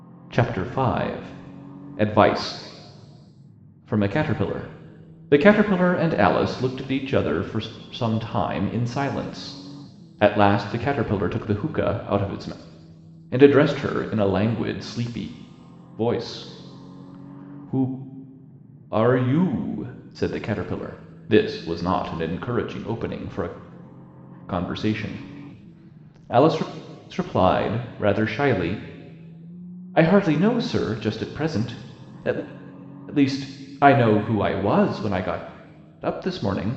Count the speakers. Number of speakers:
one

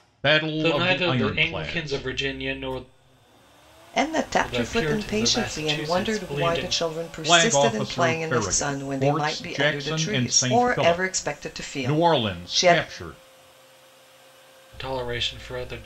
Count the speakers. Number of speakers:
three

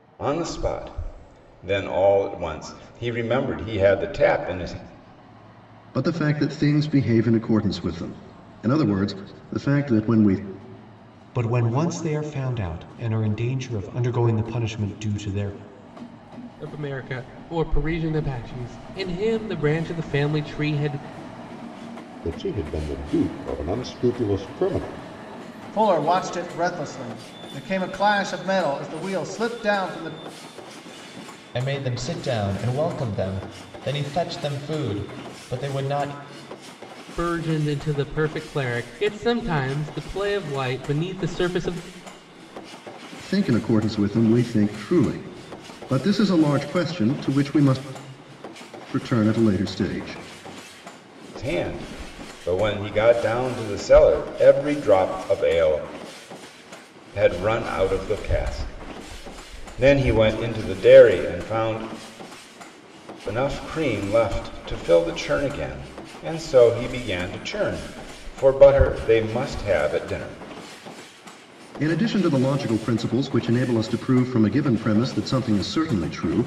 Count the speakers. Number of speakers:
seven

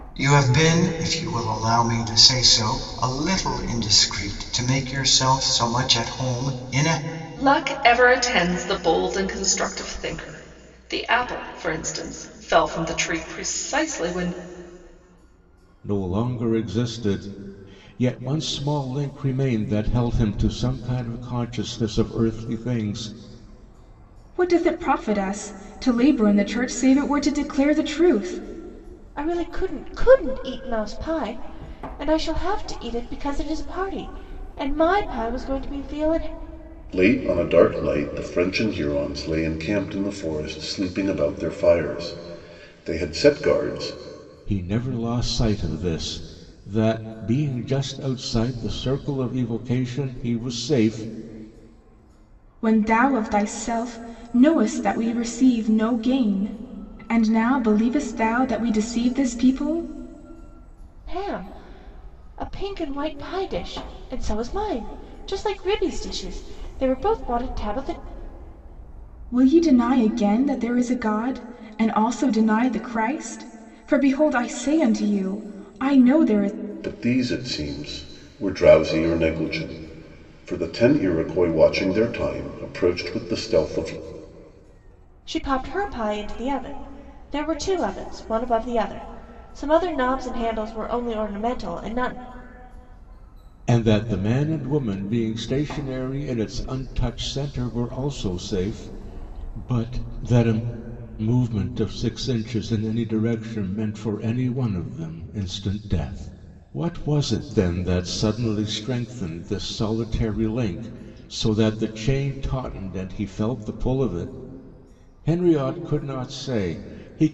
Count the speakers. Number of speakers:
six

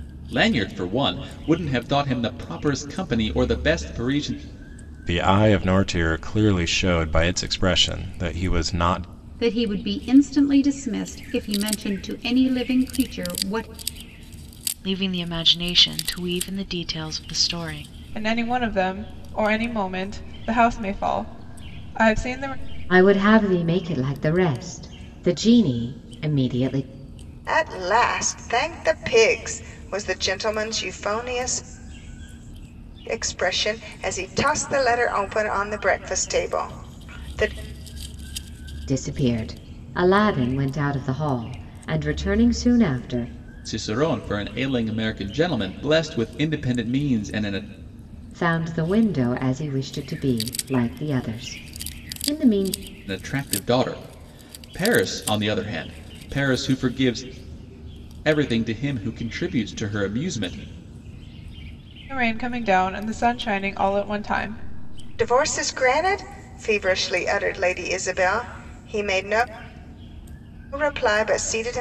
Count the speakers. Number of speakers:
seven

